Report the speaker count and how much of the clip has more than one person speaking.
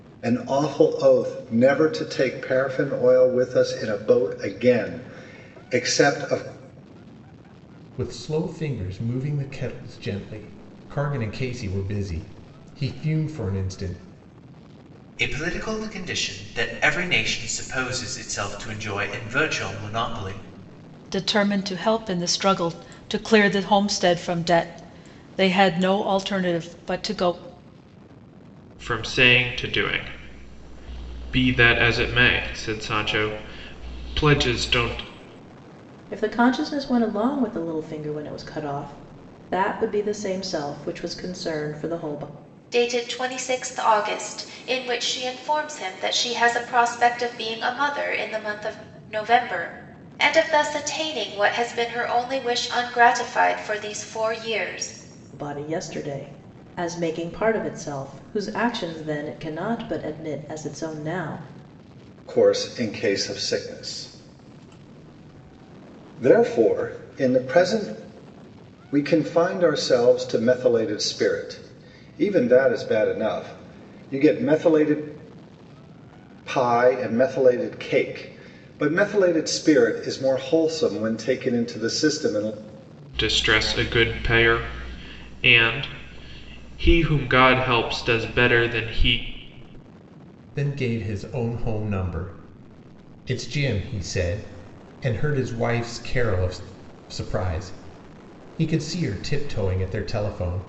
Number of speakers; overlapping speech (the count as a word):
seven, no overlap